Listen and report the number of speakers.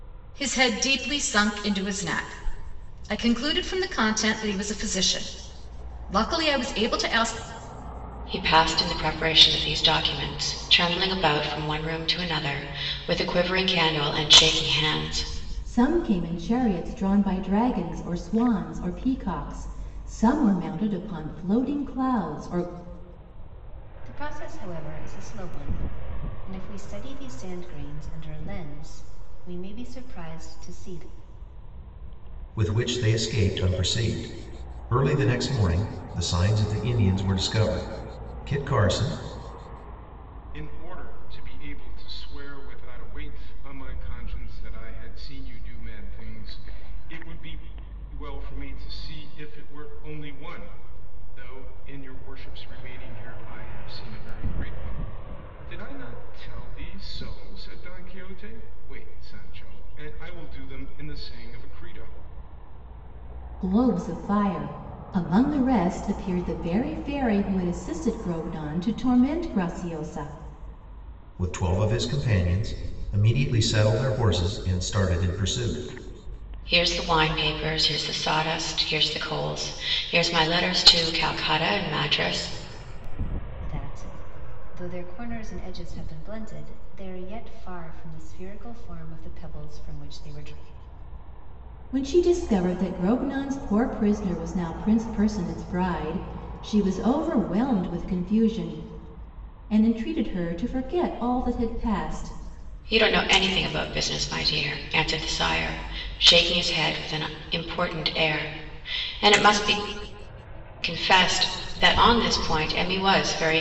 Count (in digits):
6